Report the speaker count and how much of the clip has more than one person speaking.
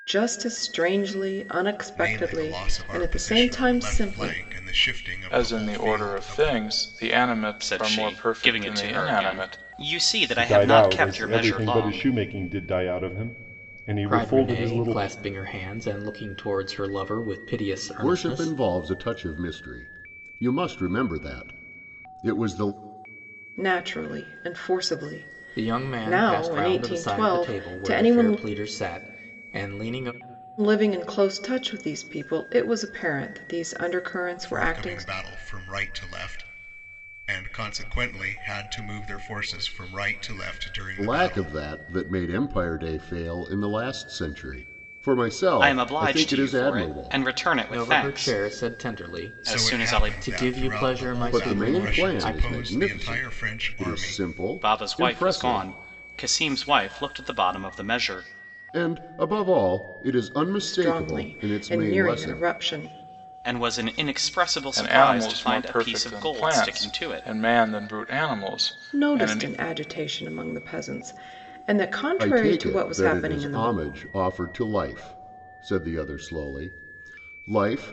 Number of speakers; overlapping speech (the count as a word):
seven, about 38%